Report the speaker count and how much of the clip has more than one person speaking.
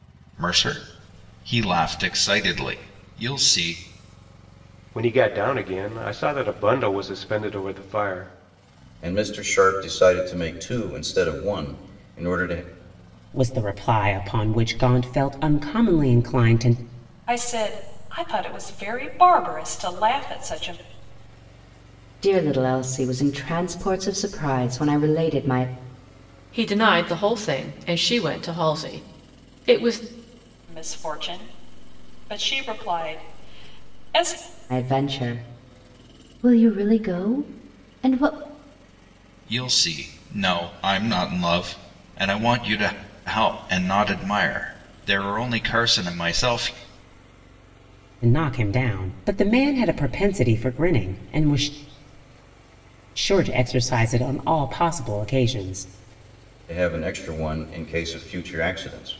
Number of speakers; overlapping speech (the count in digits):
7, no overlap